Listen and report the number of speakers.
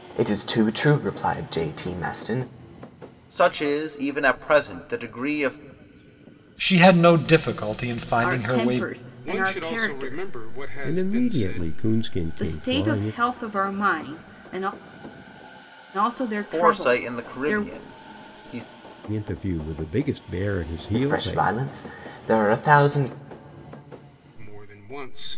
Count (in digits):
6